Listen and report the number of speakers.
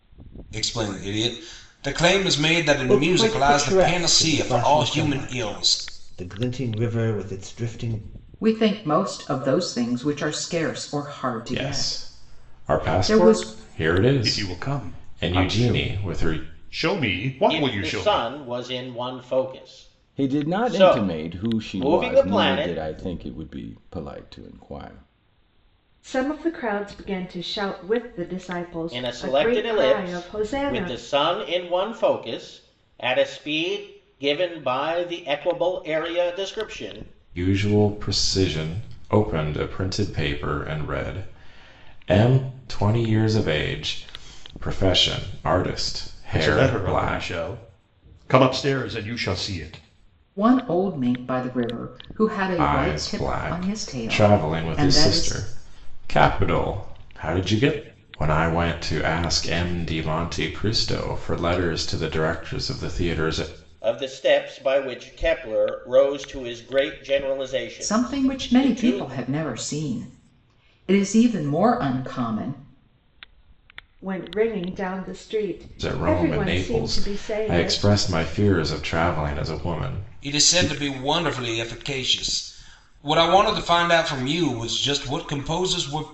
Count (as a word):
eight